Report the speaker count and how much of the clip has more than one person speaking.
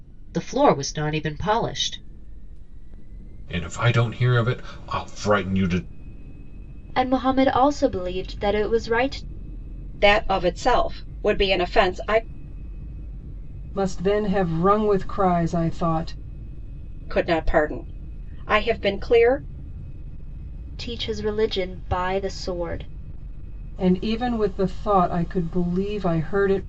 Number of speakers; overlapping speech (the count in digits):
5, no overlap